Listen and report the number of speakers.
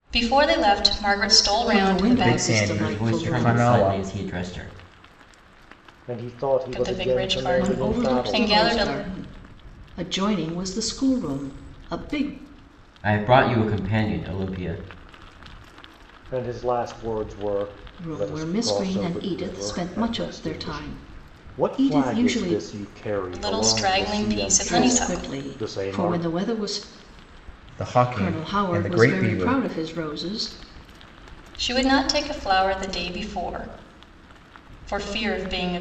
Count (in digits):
5